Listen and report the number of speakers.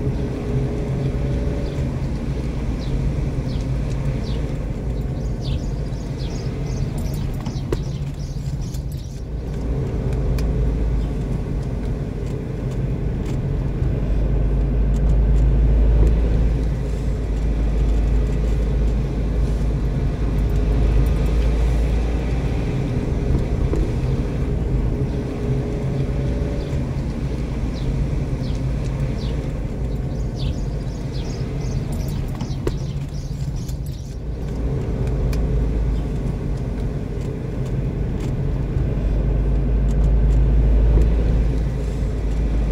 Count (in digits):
0